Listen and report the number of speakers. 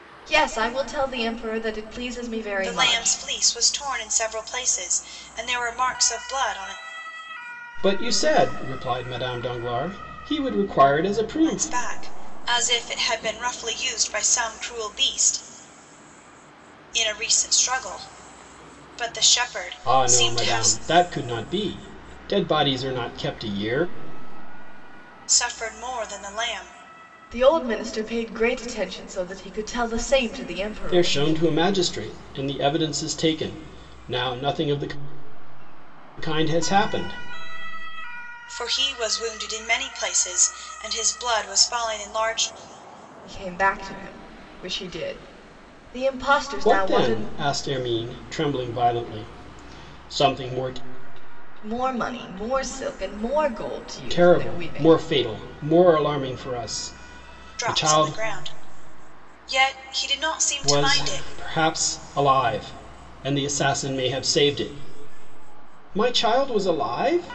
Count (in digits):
3